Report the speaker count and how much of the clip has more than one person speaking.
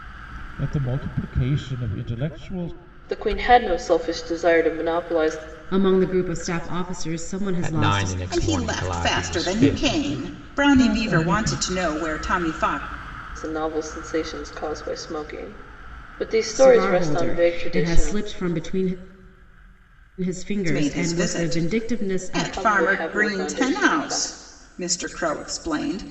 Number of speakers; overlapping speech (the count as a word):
five, about 36%